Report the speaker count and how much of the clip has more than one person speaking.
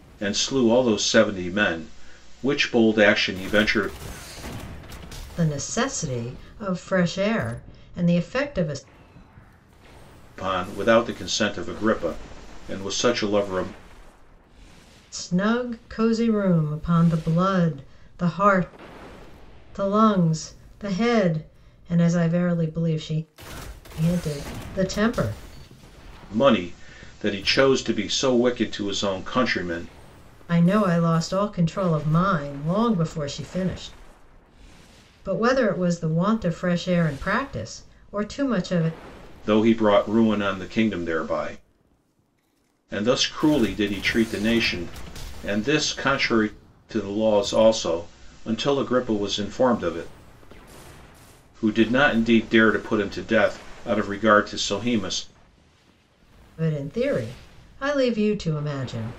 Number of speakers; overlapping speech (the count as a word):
two, no overlap